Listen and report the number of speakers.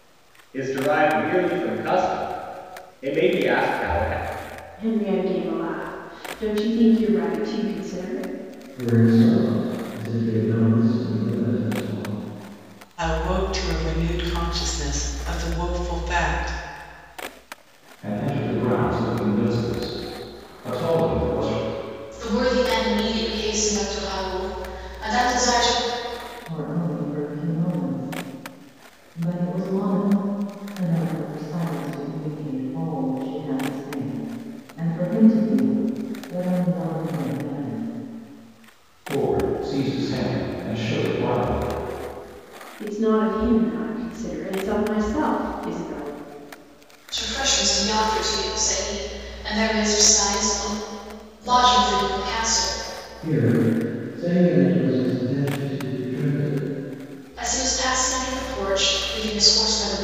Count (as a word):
seven